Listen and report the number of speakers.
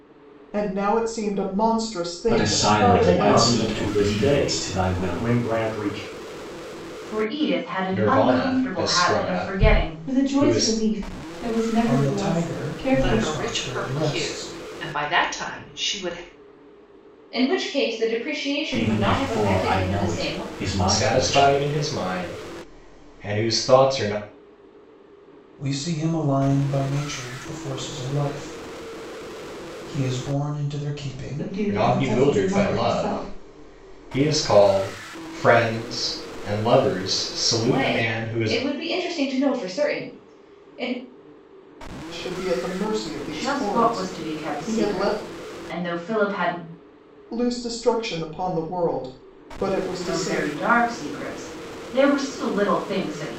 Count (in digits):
9